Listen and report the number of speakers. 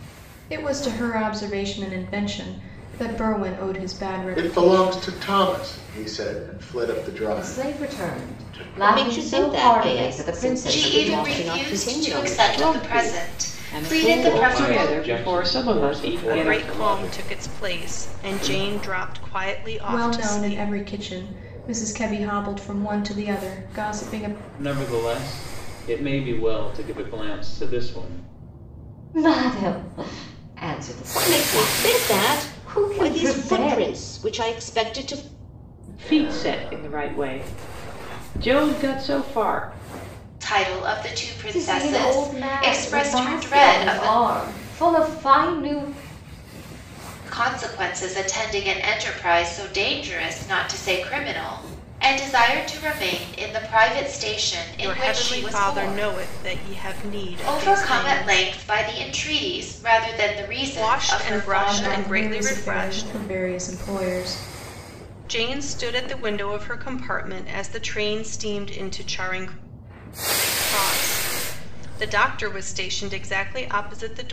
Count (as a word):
eight